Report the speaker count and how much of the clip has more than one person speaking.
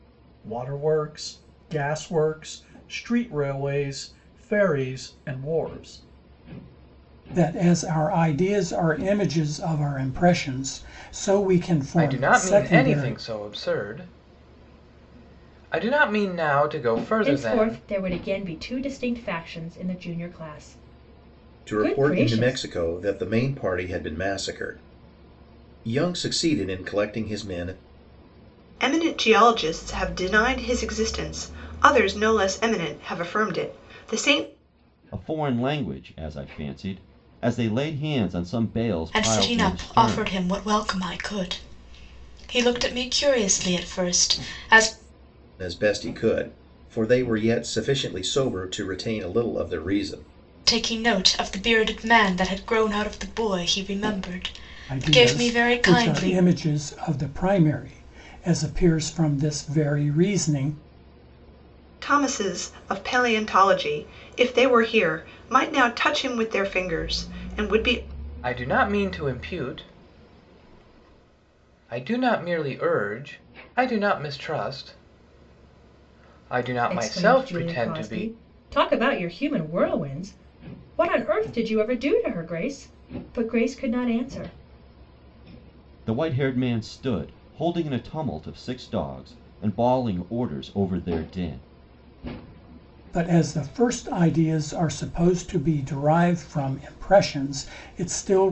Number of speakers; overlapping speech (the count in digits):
8, about 7%